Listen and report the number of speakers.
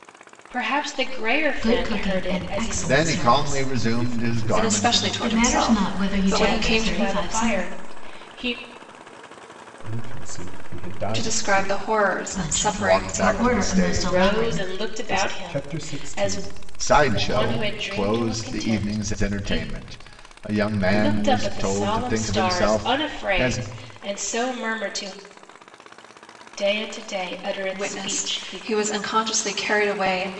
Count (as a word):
six